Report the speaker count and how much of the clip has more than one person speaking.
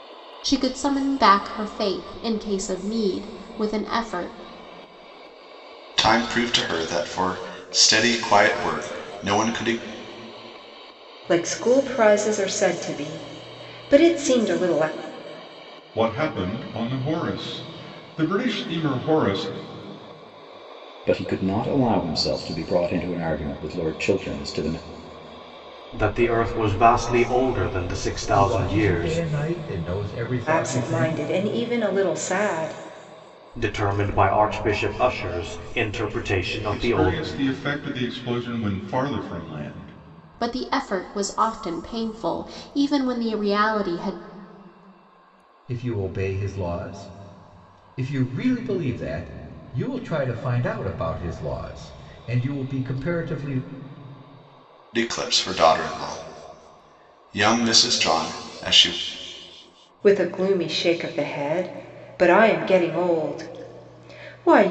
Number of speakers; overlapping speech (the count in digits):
7, about 4%